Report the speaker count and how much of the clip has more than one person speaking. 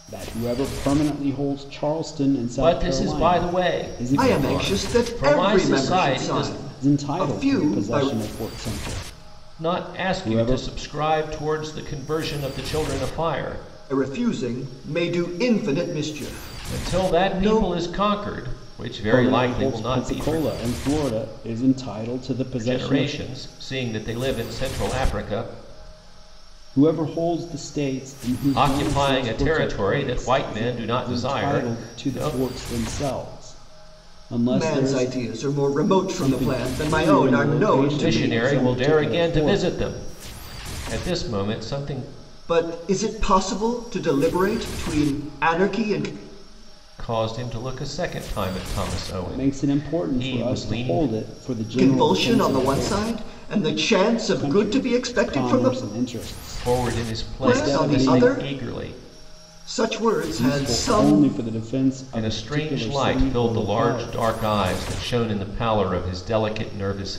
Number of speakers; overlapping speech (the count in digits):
3, about 41%